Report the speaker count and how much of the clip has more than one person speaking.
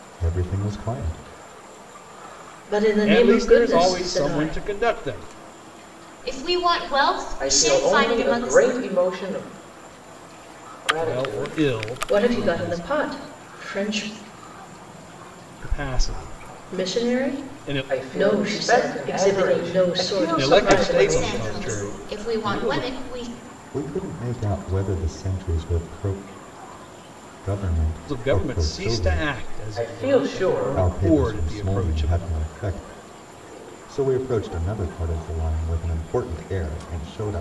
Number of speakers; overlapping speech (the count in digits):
5, about 38%